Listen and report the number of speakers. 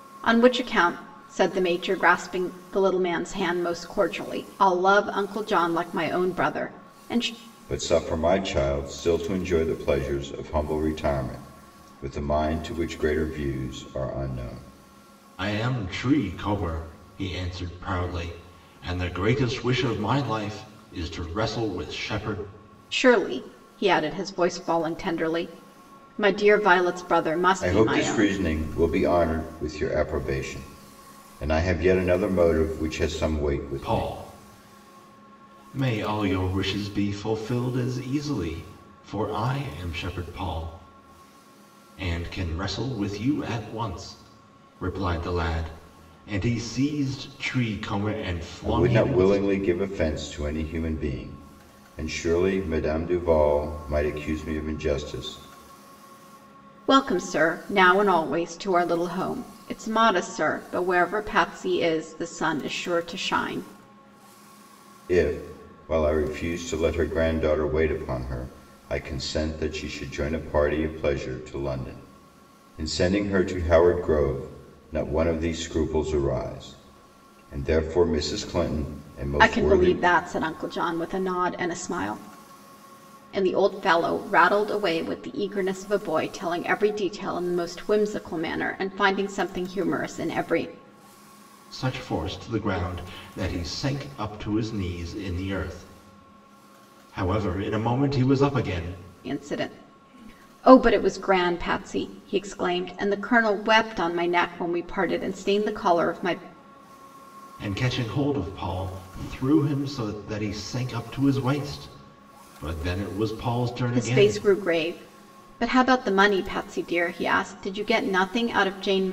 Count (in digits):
3